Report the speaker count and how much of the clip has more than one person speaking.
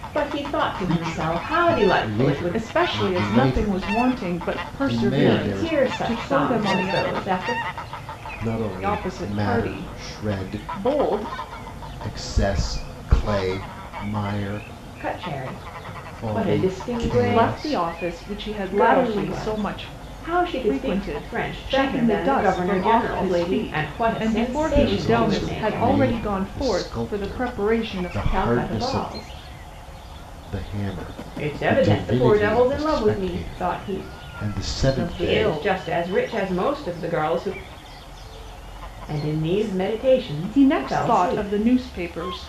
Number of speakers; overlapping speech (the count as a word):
three, about 56%